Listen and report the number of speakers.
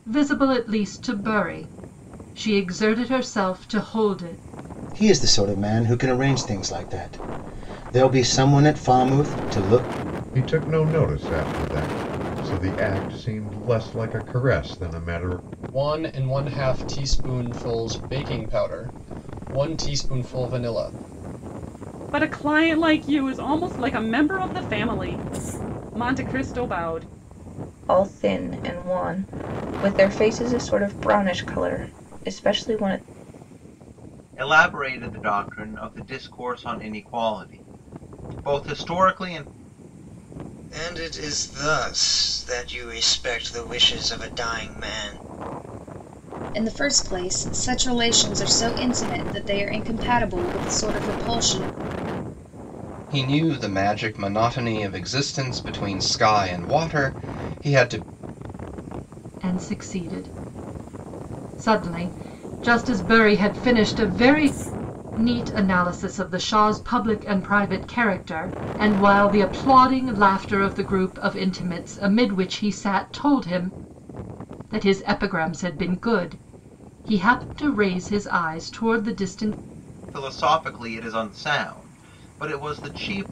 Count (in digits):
10